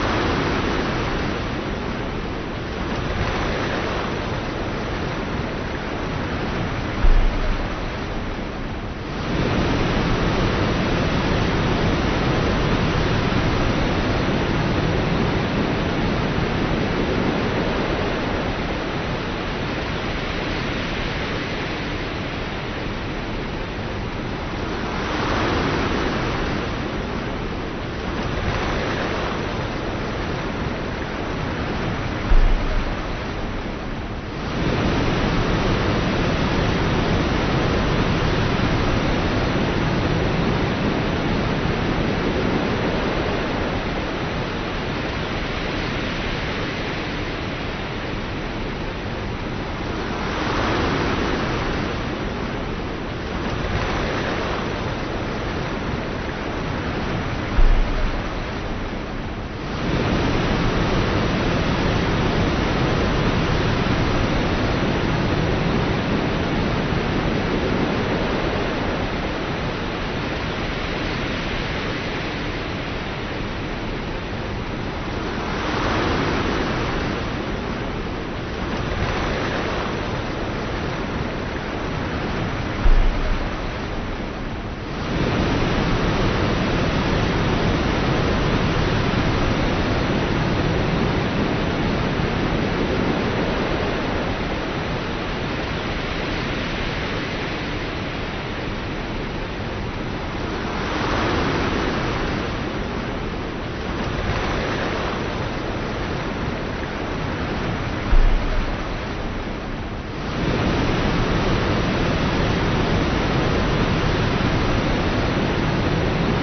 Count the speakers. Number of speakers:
zero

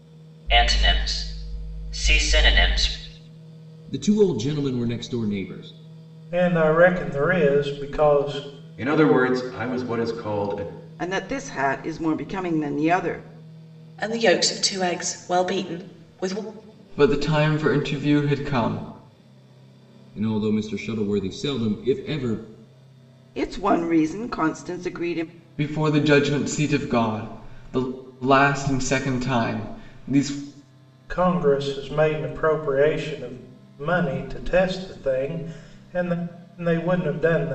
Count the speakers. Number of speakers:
seven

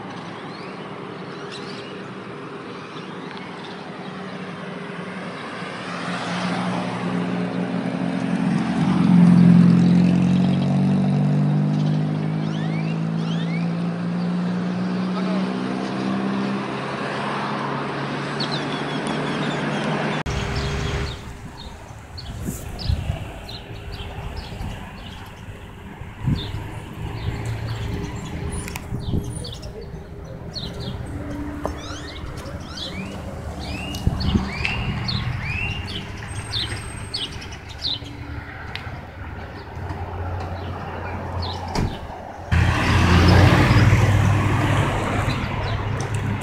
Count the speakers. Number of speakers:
zero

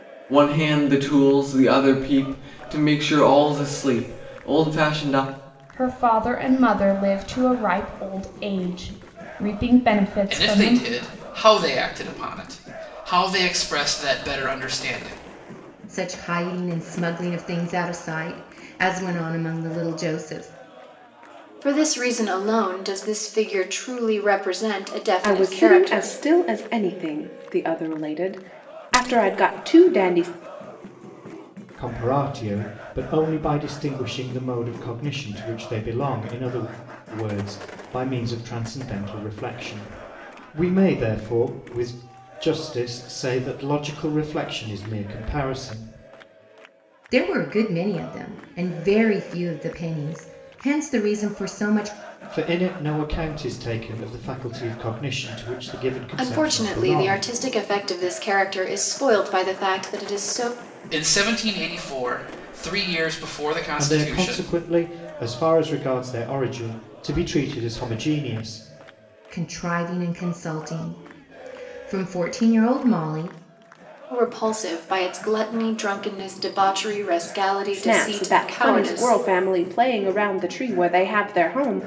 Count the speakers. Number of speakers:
seven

